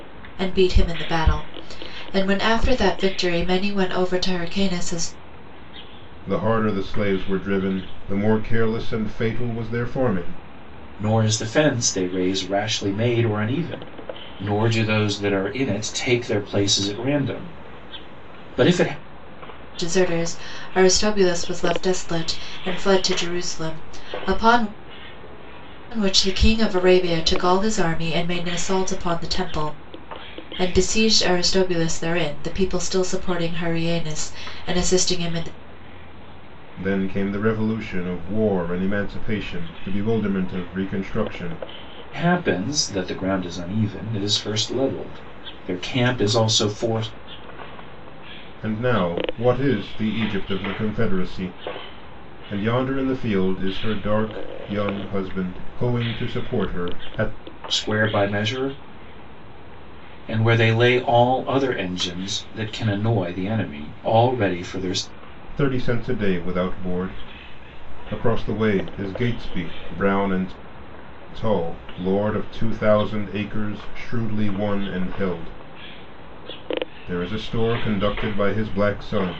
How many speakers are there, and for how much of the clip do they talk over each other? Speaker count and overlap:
3, no overlap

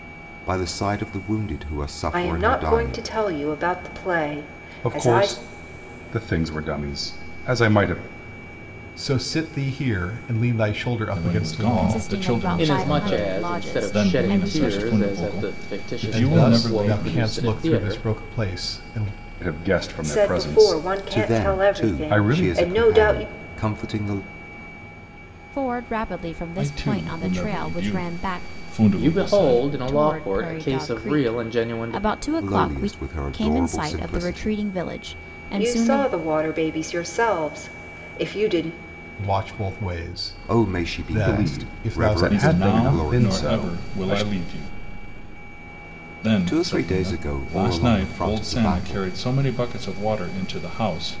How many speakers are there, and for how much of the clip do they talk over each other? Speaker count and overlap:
7, about 49%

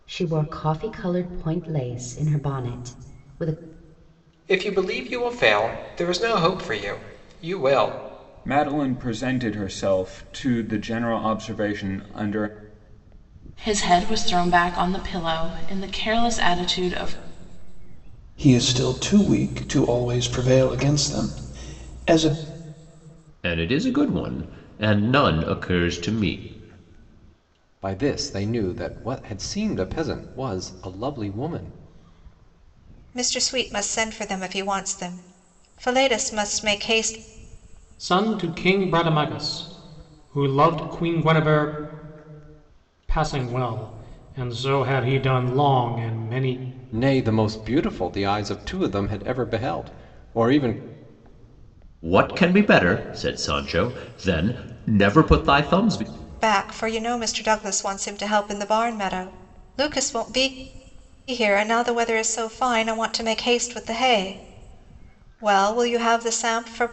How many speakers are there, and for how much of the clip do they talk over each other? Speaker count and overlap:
9, no overlap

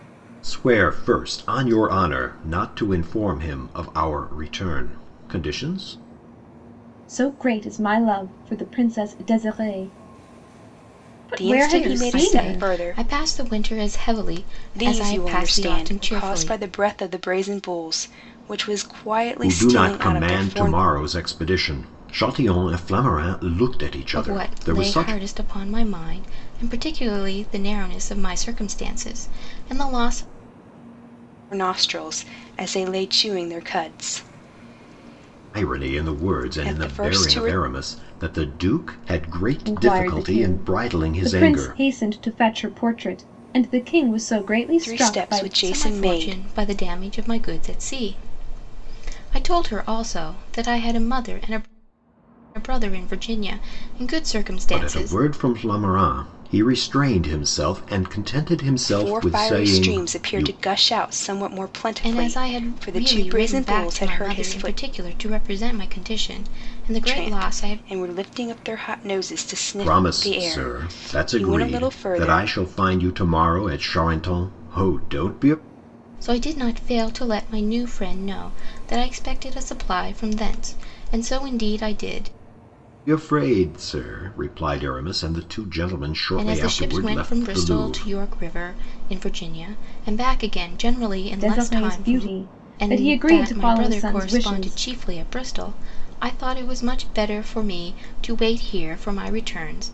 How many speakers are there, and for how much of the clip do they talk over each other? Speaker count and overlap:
4, about 26%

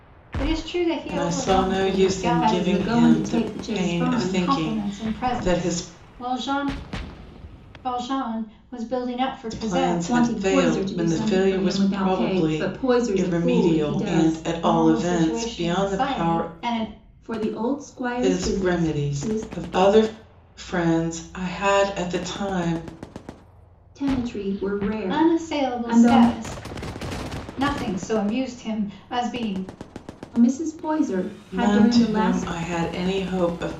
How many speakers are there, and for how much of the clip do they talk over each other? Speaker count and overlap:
3, about 45%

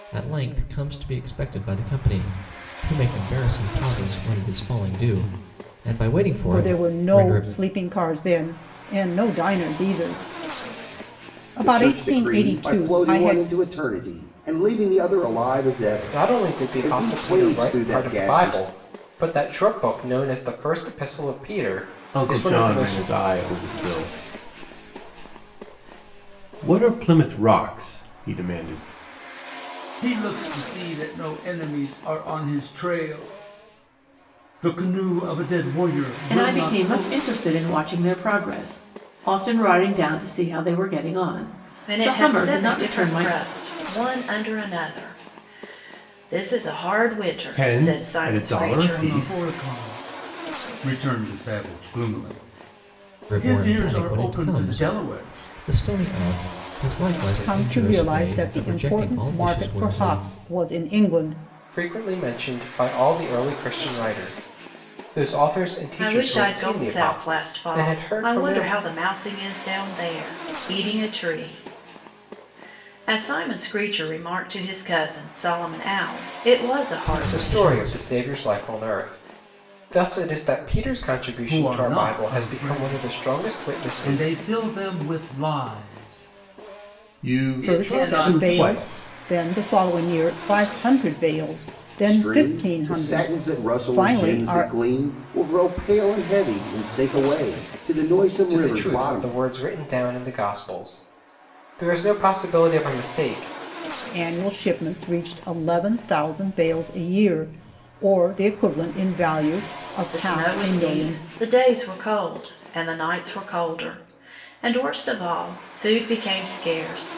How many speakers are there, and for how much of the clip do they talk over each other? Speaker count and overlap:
8, about 25%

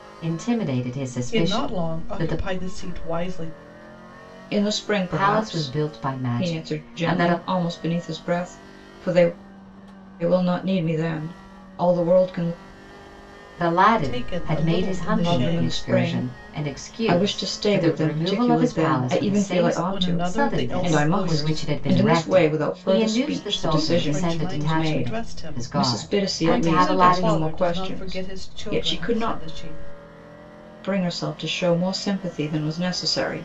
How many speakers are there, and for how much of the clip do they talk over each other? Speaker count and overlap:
3, about 54%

